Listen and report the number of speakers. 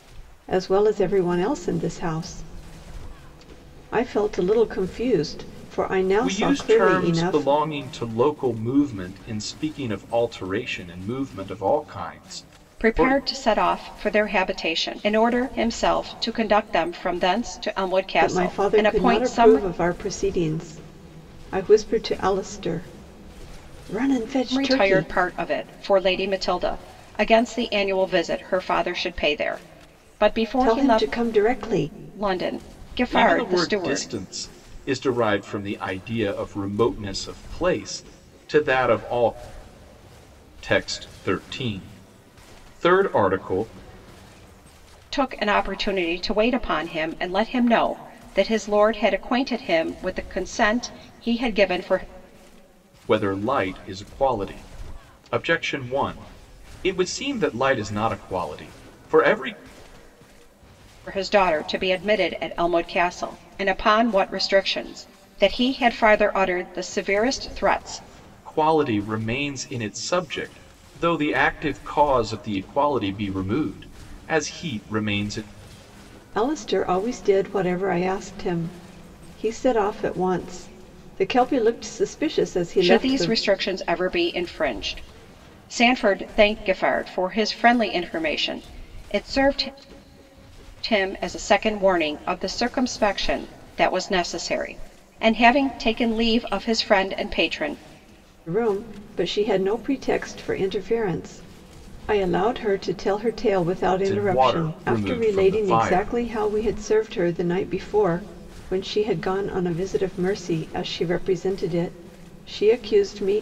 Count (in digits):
3